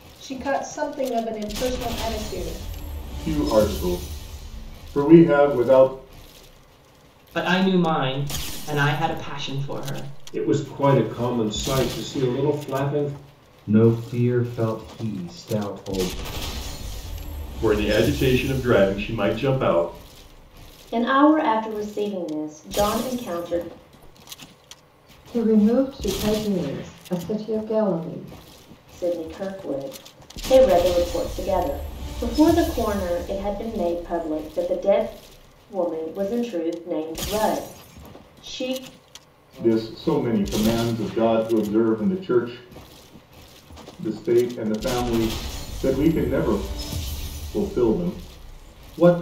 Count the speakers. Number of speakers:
eight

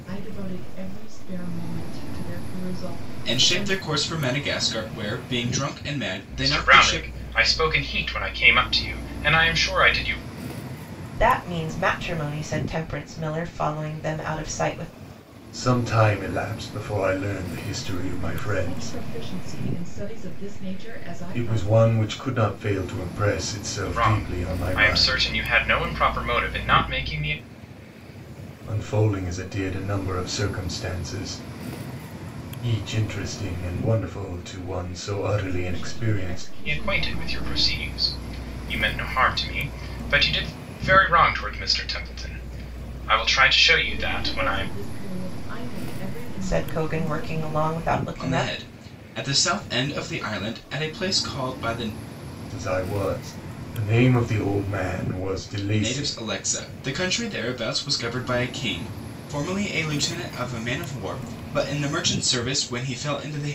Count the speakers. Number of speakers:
five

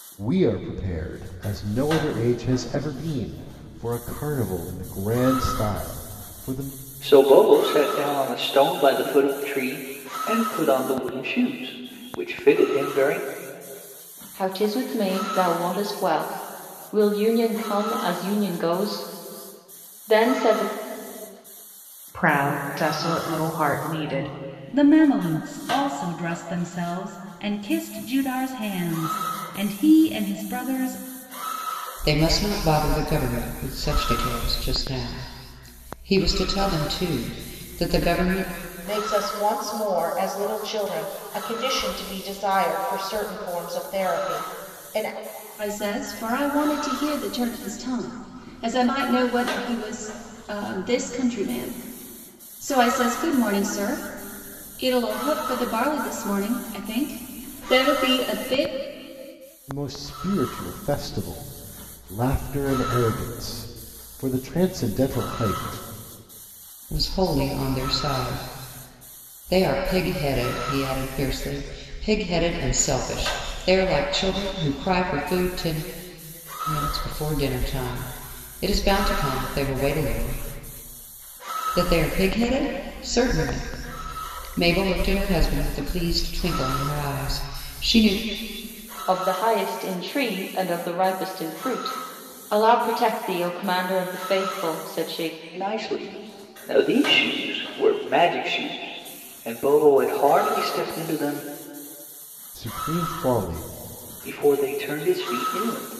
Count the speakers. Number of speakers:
eight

